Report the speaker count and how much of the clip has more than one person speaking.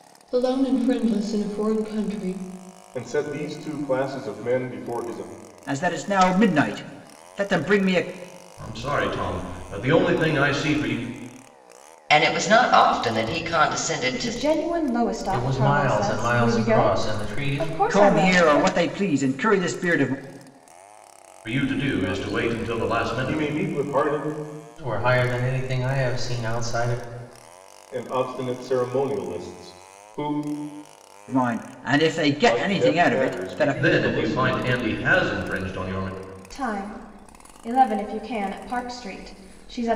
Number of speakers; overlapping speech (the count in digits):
7, about 19%